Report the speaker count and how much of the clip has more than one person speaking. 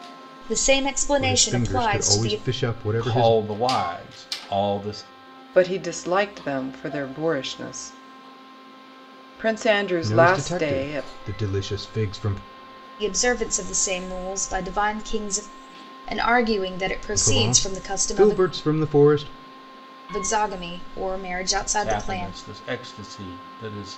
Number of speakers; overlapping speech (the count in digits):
4, about 19%